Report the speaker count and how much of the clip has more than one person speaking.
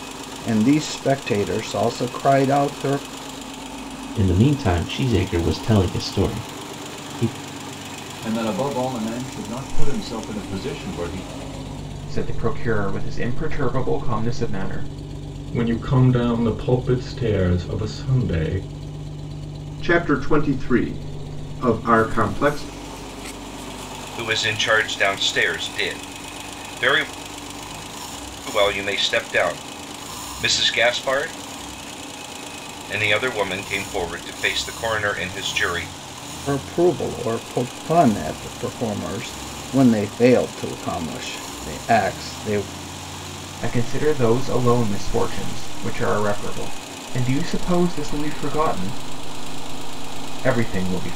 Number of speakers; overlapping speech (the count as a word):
seven, no overlap